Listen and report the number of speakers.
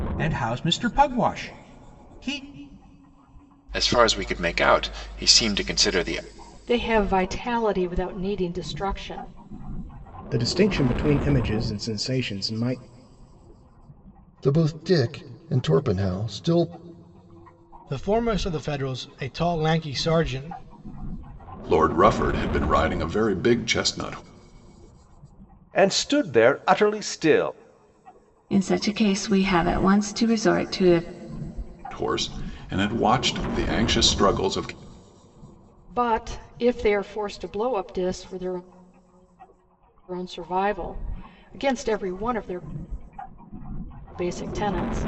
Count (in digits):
9